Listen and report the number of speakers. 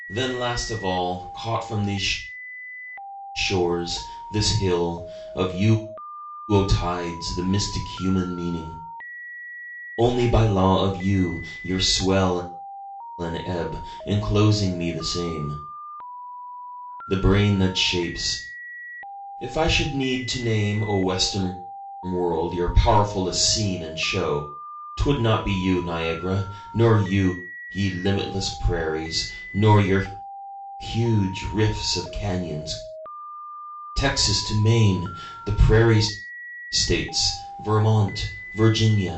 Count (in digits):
1